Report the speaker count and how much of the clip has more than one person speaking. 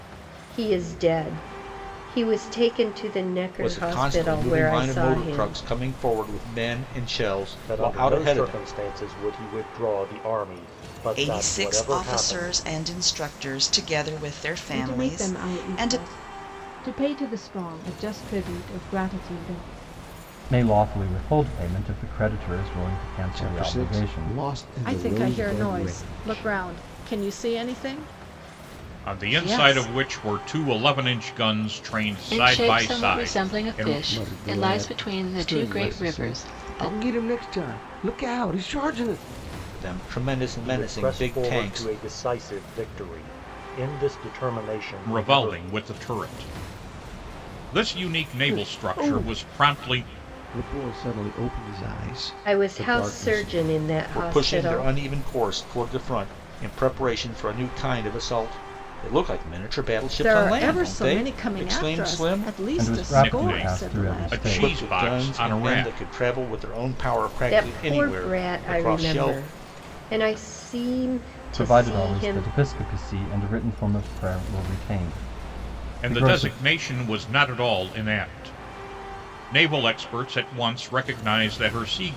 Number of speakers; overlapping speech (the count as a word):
ten, about 35%